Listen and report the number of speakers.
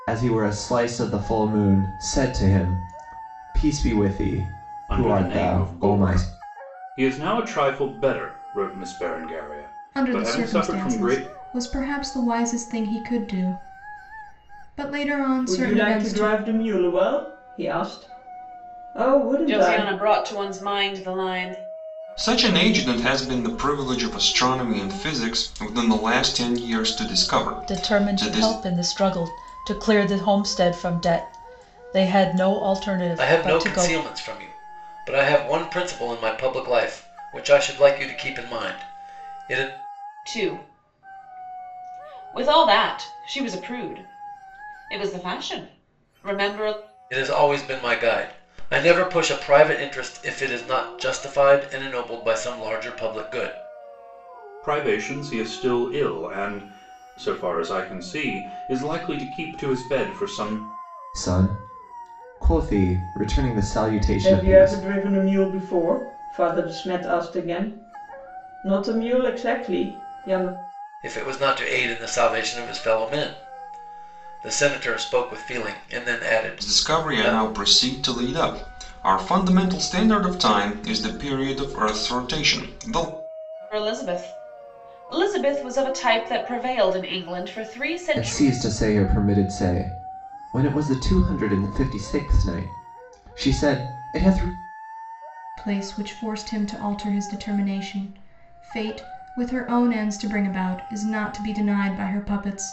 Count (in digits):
8